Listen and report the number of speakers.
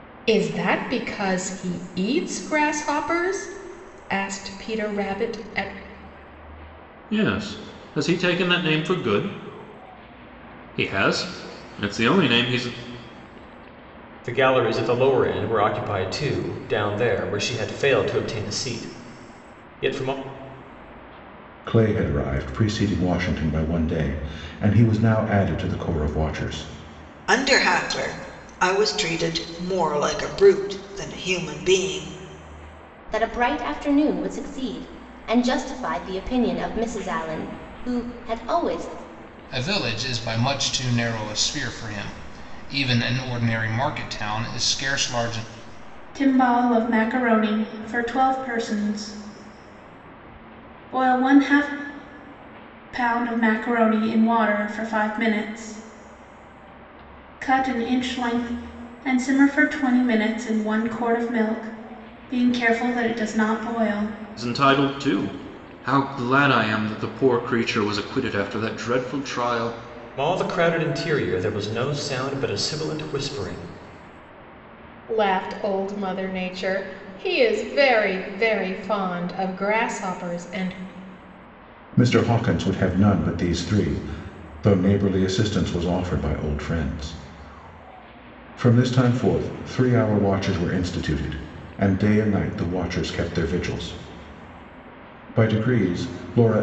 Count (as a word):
eight